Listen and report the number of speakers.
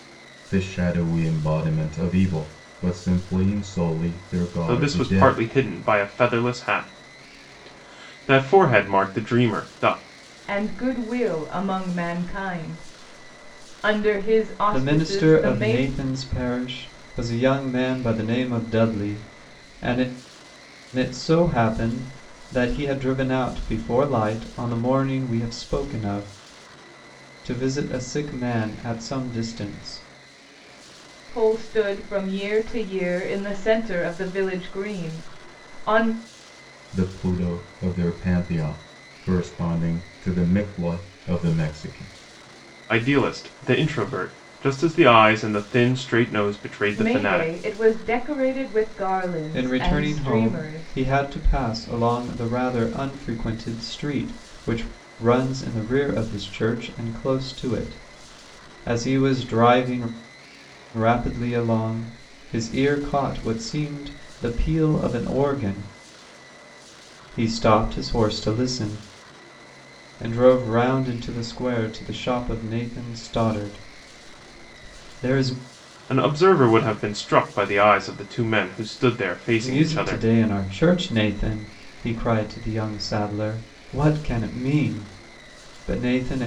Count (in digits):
4